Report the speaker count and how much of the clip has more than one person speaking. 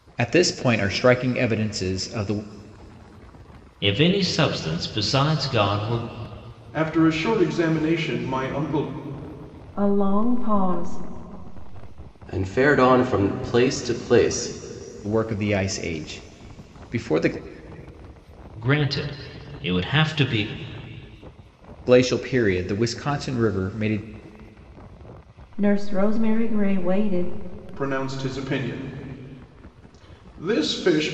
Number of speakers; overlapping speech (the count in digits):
5, no overlap